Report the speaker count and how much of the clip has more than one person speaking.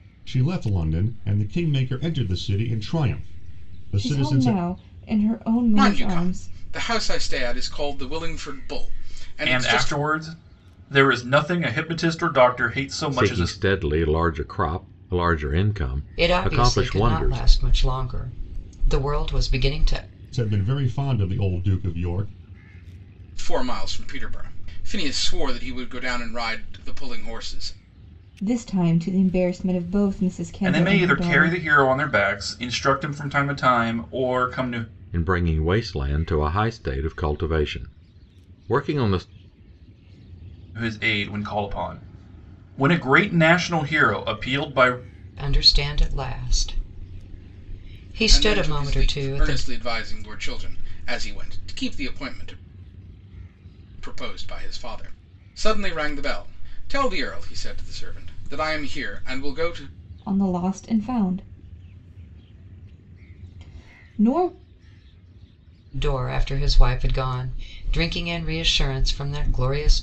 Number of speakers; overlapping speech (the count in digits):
6, about 9%